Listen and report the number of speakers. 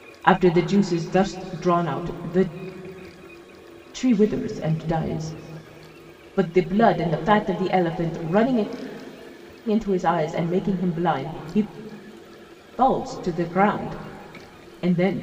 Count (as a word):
one